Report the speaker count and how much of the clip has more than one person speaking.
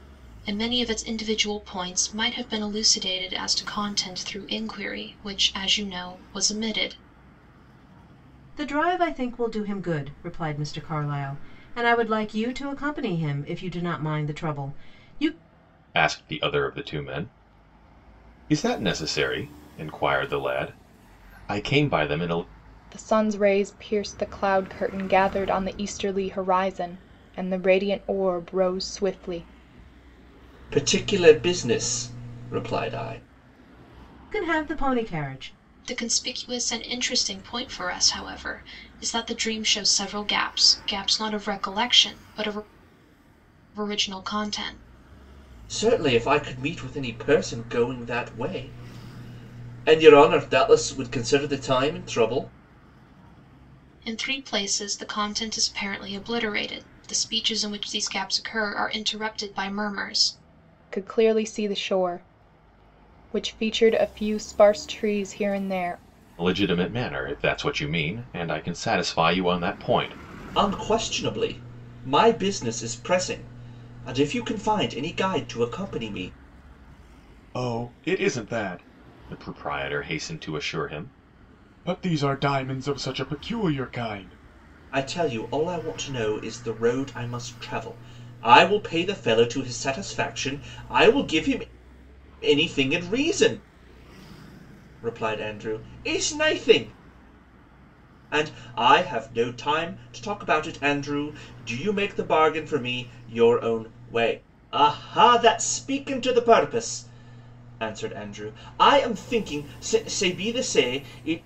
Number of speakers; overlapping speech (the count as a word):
five, no overlap